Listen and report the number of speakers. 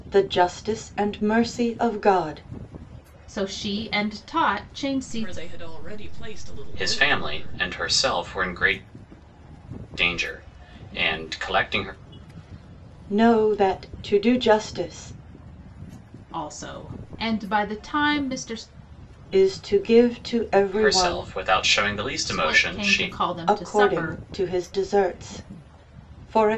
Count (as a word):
four